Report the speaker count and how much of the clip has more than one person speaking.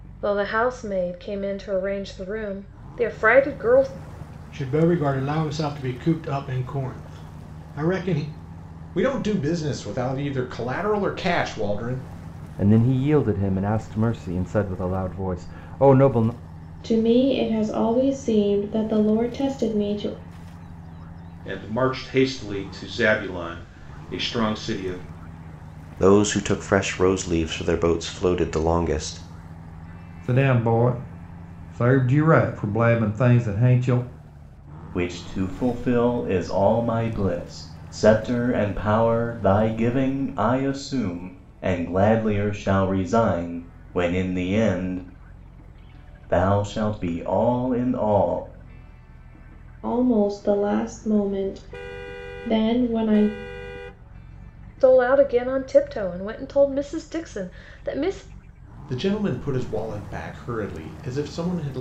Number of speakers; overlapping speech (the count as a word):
nine, no overlap